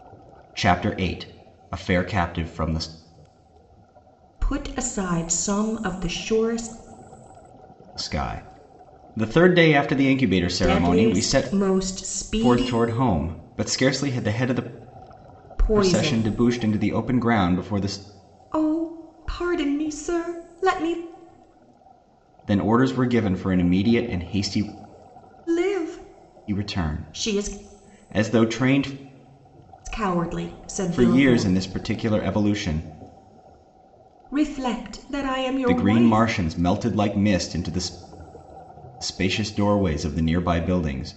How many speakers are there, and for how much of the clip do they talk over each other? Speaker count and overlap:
2, about 11%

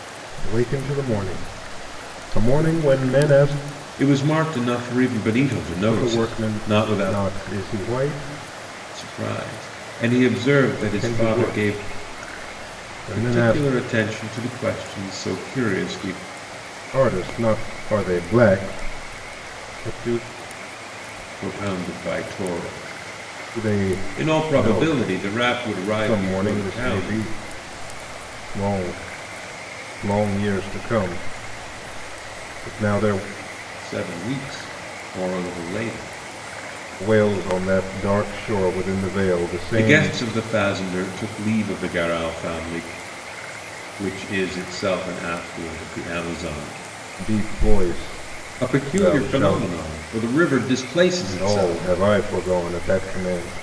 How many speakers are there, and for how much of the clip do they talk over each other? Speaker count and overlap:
2, about 14%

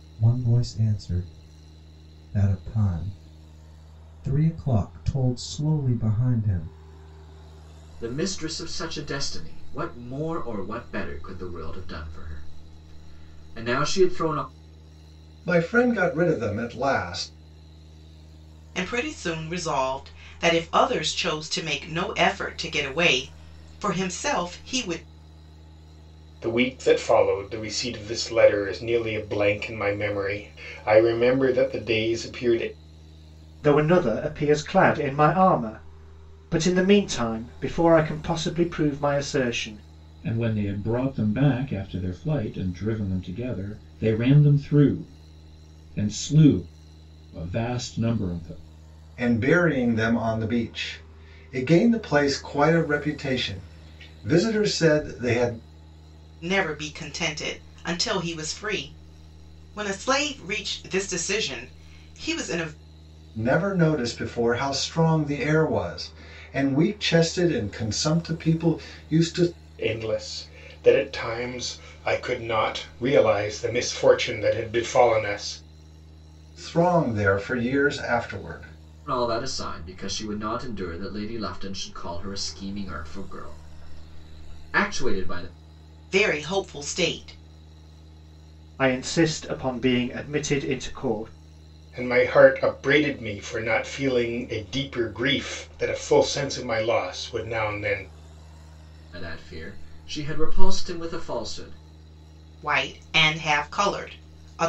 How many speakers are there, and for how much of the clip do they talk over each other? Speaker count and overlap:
7, no overlap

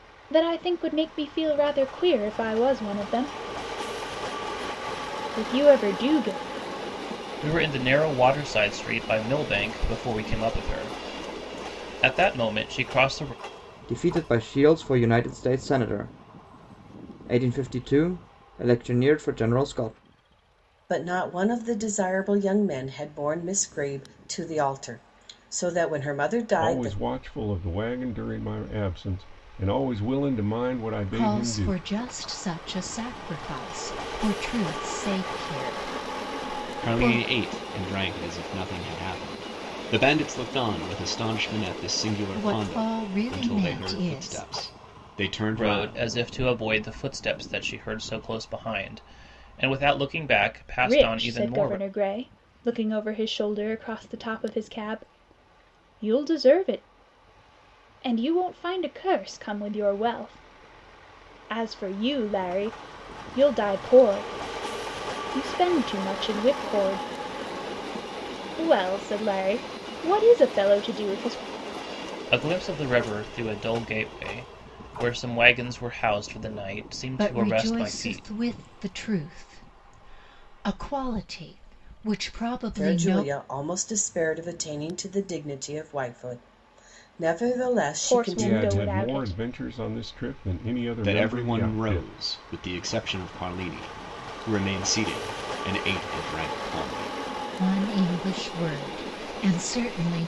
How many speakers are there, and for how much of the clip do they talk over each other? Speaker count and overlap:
7, about 9%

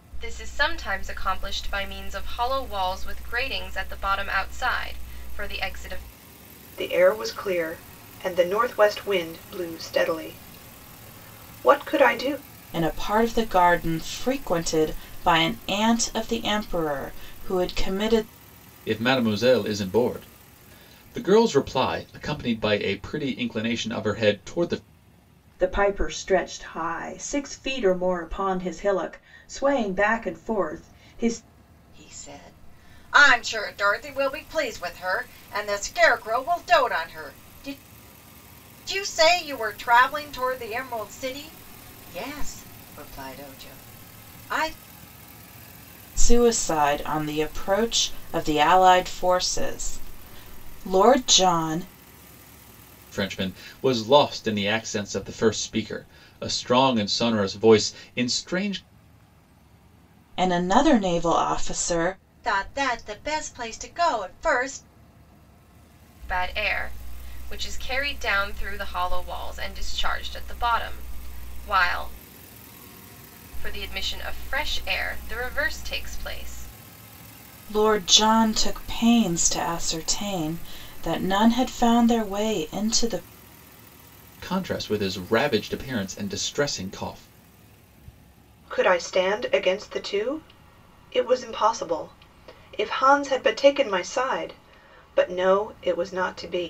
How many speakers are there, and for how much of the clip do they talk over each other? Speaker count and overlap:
6, no overlap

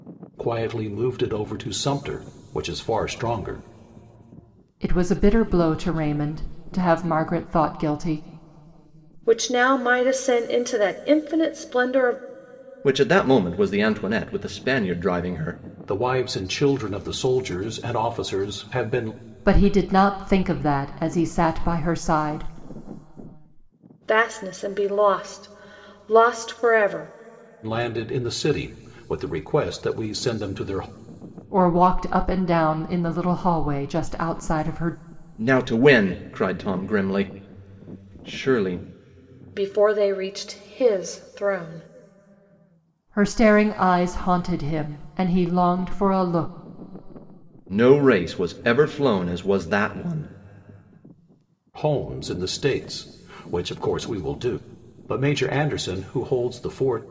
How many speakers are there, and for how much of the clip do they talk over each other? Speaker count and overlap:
4, no overlap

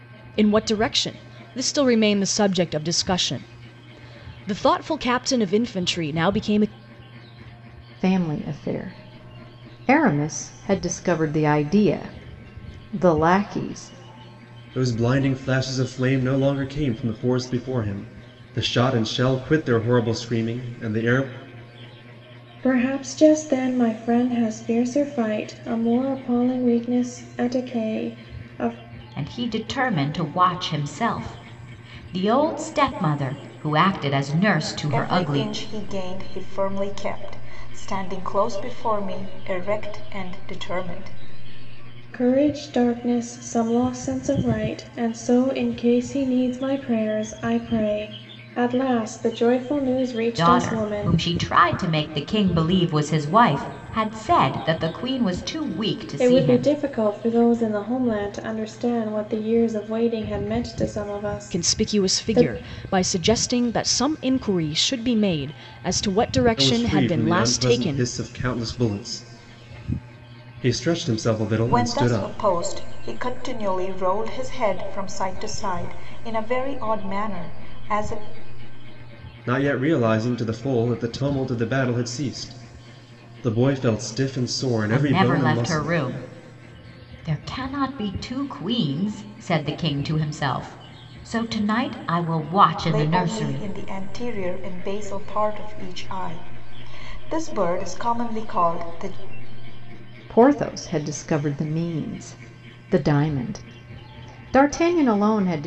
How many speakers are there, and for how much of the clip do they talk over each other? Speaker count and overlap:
6, about 7%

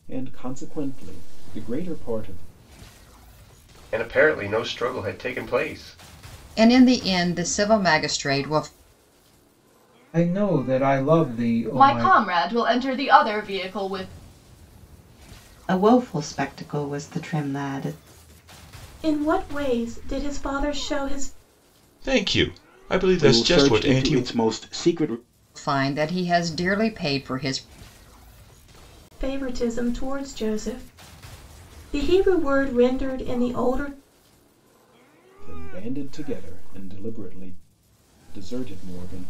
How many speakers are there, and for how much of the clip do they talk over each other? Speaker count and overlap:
9, about 4%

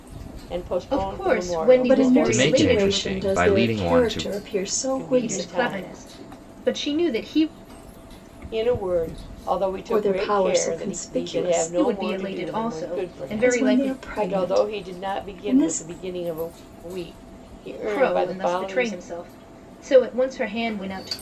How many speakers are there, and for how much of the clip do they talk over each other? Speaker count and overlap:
4, about 54%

